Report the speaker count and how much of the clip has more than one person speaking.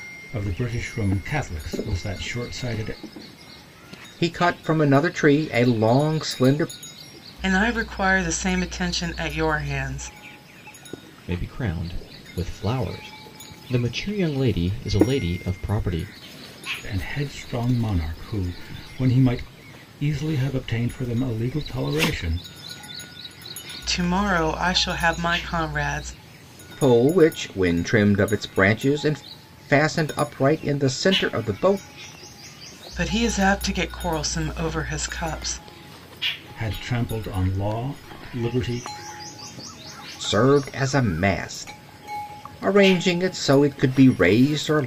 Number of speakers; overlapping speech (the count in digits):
4, no overlap